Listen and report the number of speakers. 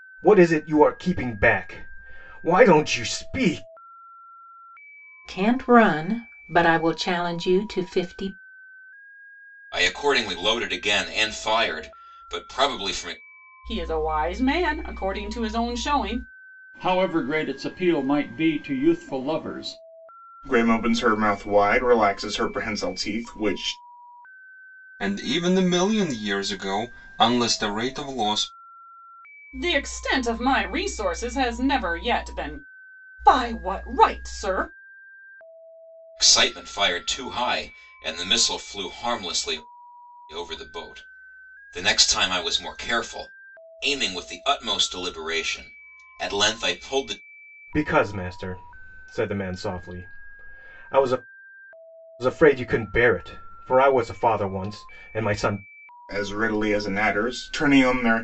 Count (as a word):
seven